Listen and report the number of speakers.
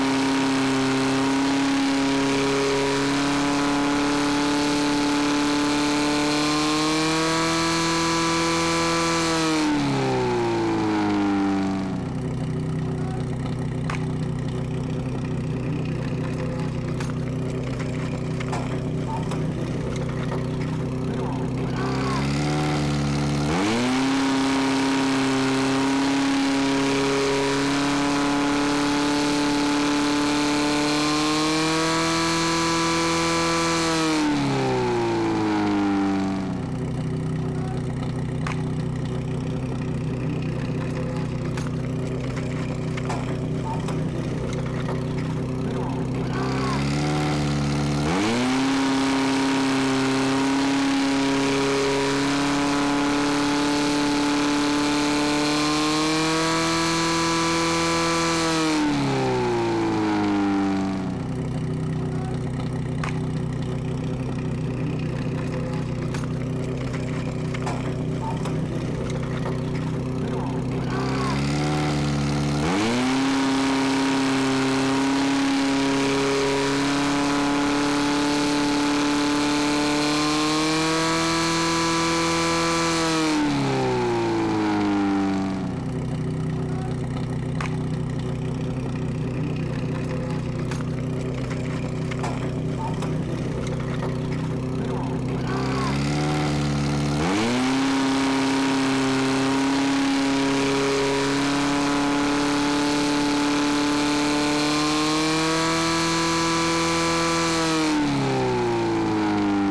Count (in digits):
0